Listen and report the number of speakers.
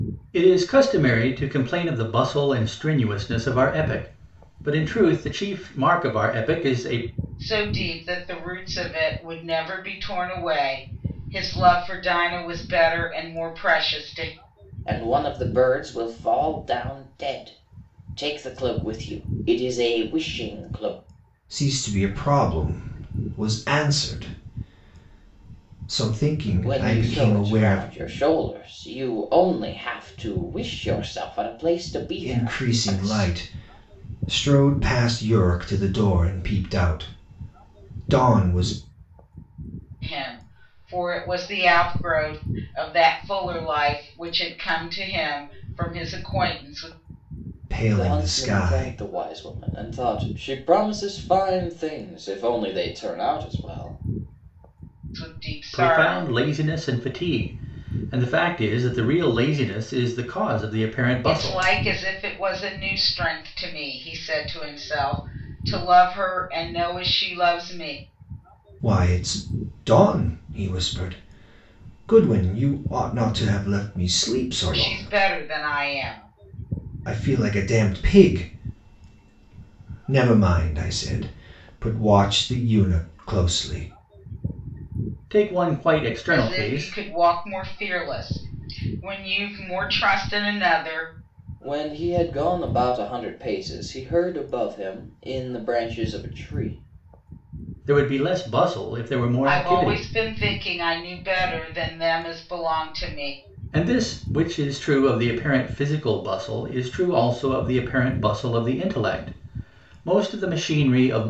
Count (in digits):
4